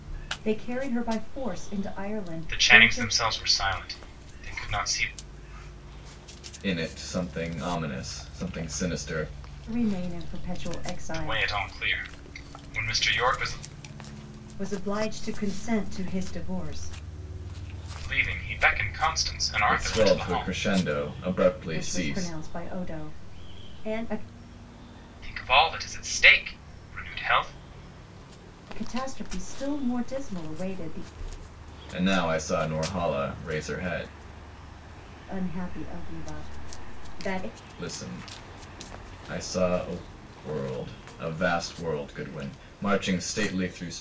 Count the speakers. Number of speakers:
3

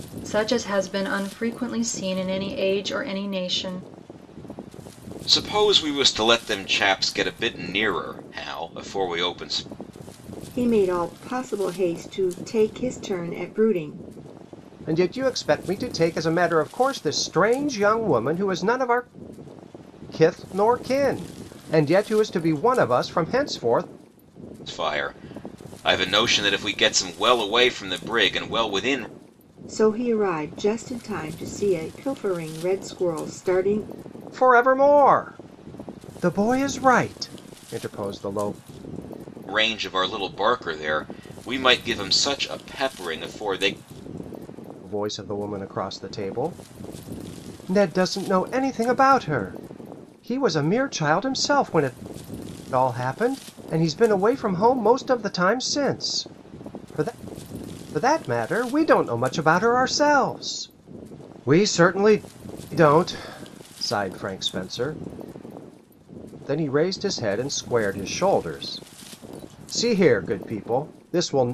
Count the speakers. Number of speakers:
4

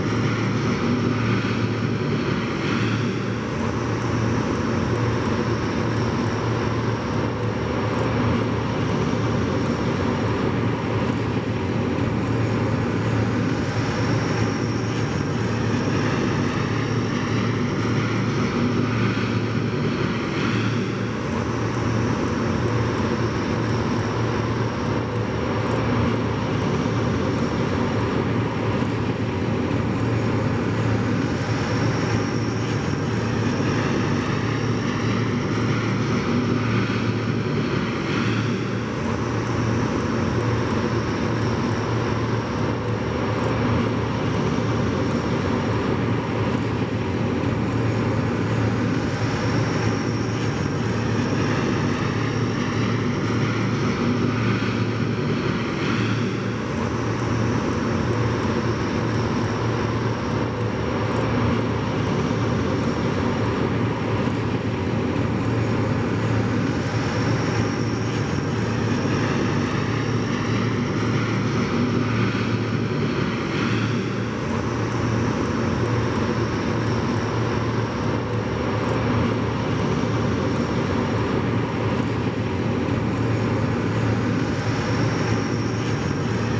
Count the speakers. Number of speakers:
0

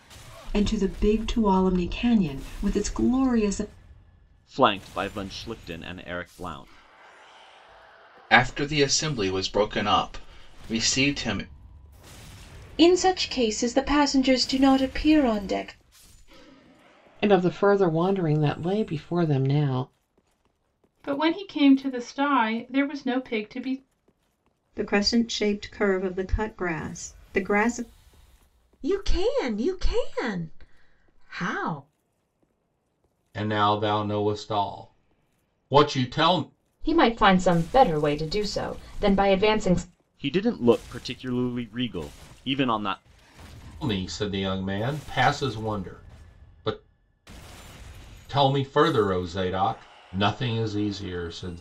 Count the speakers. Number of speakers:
10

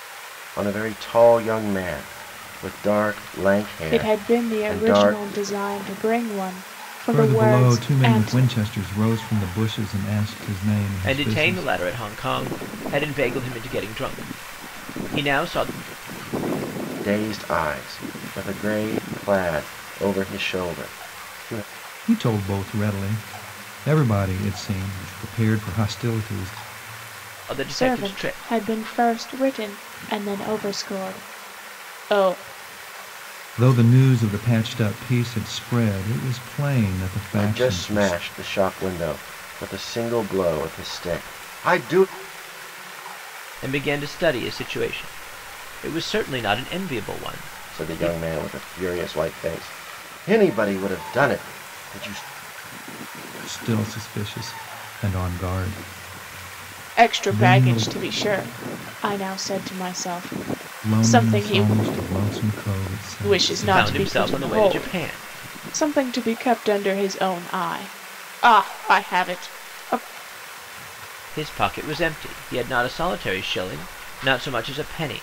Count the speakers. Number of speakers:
4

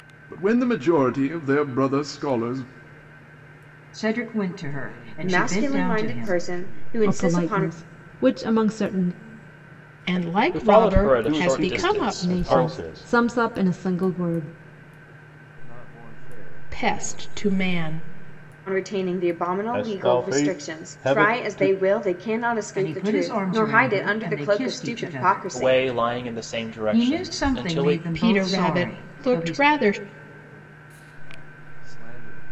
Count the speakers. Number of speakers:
8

